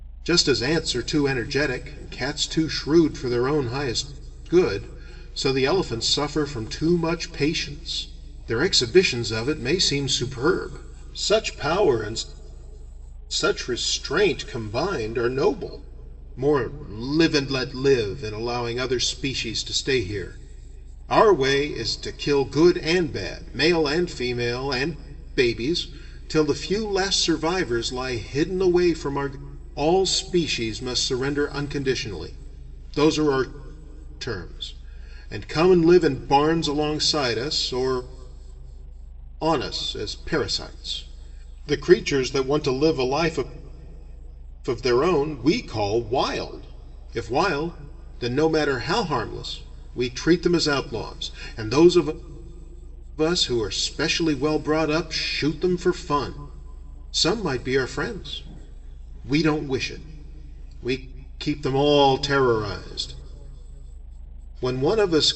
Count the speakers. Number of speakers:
1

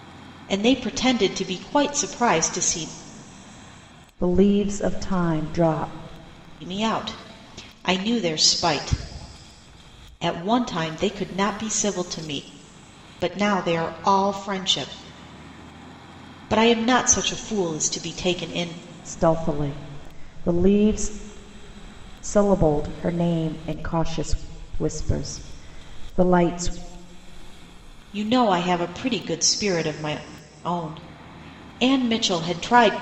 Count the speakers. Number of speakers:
2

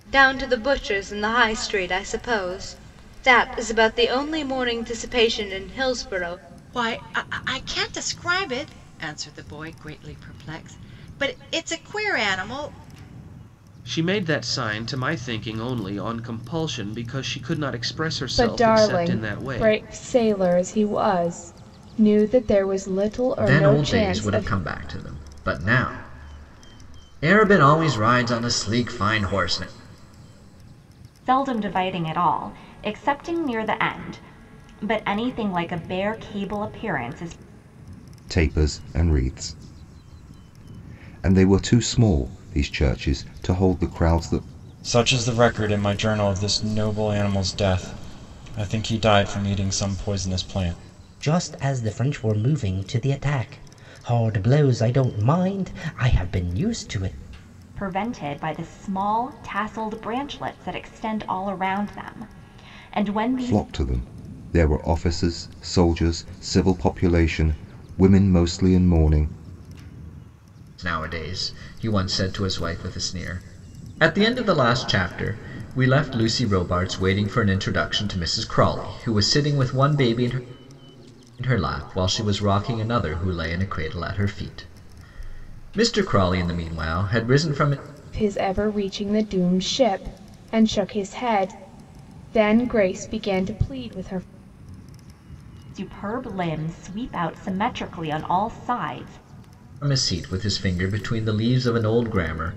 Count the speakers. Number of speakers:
9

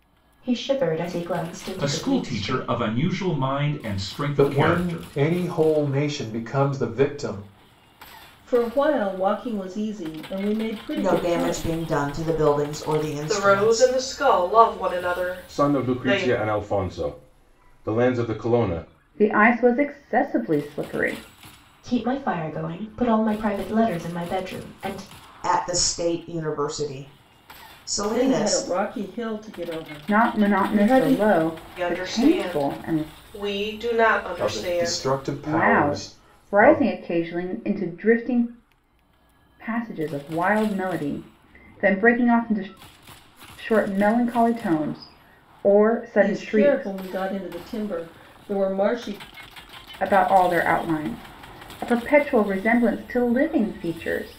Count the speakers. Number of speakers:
8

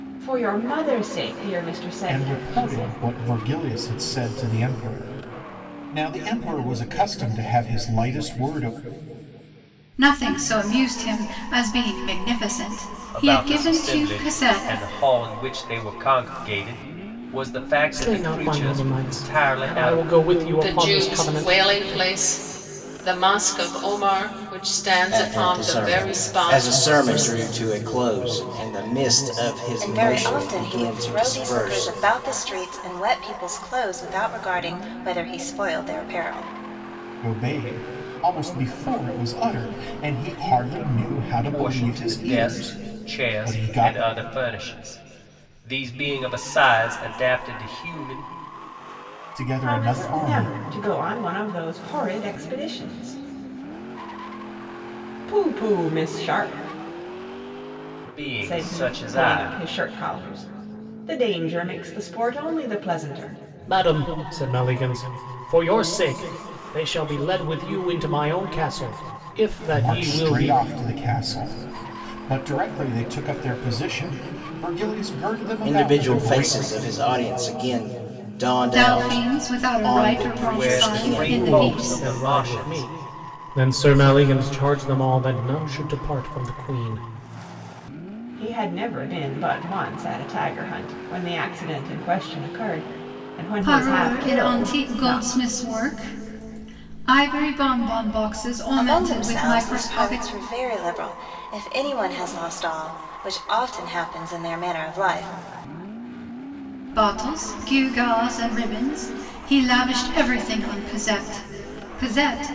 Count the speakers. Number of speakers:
8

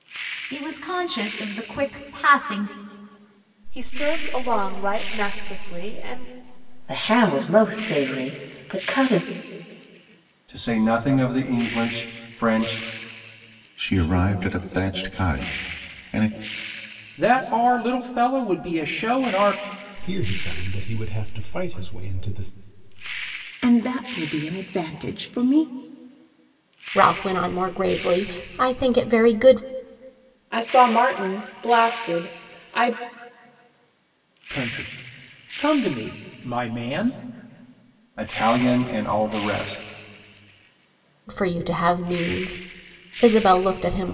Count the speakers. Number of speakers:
10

